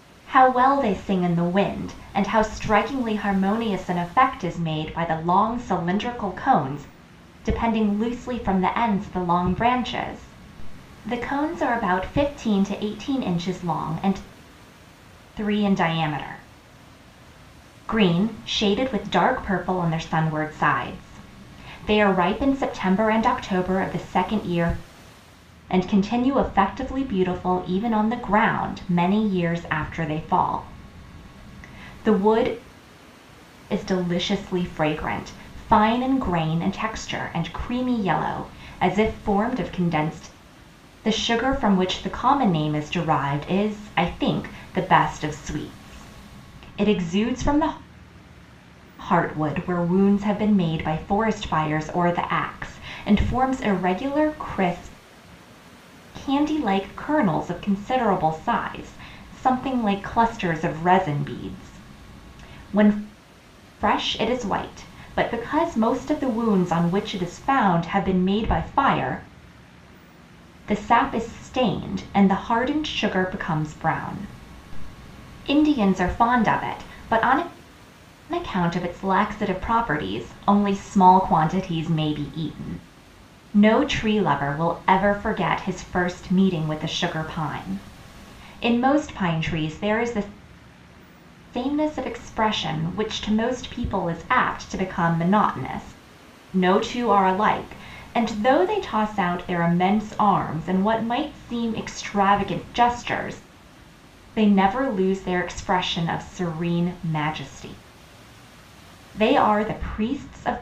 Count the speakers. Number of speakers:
1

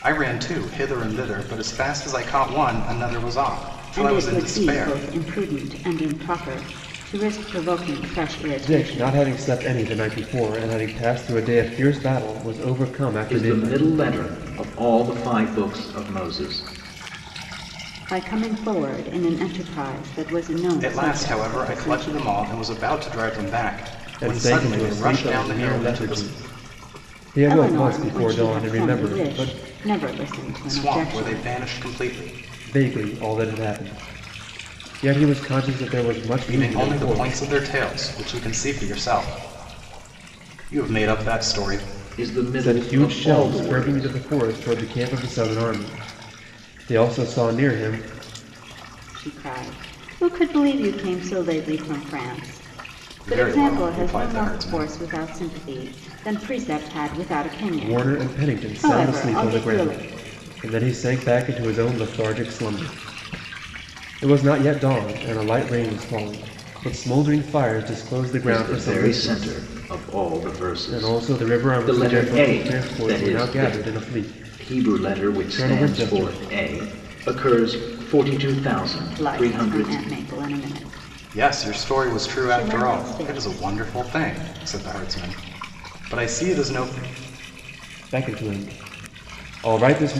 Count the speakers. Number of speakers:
4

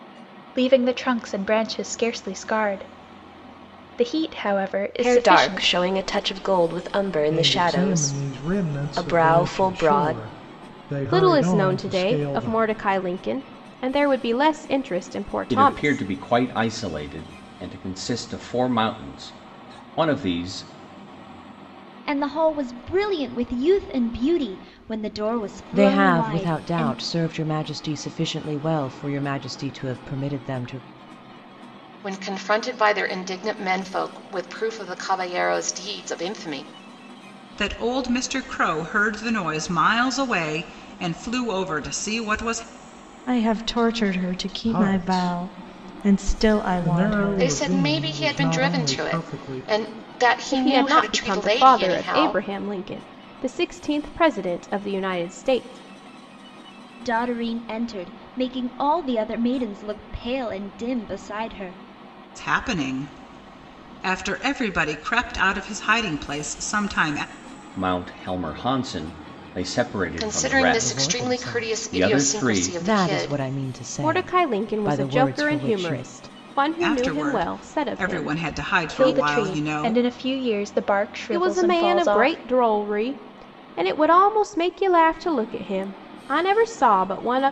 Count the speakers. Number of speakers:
10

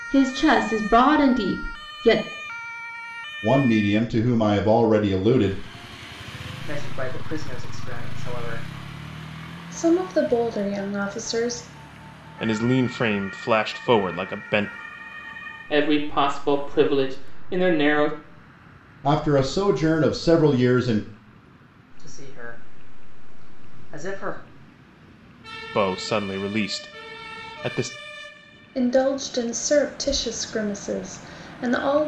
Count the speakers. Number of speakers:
6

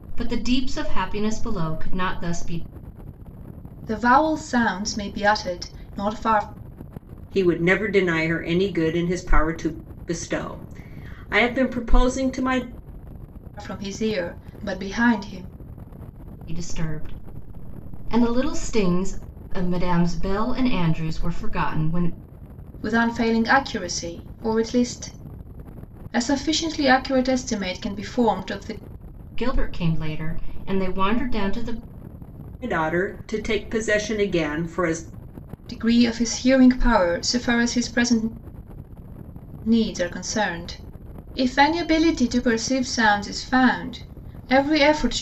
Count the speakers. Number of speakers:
3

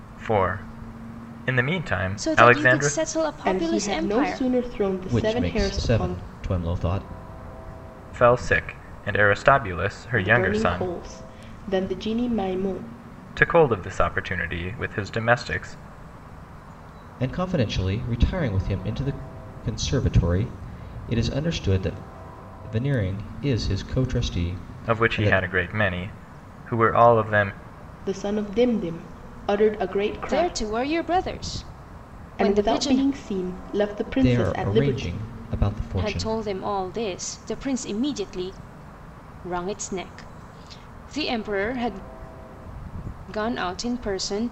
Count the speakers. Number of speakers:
4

